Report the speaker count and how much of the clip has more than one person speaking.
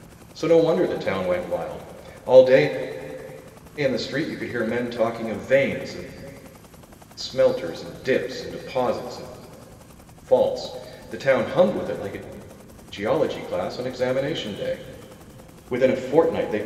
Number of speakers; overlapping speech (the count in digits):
1, no overlap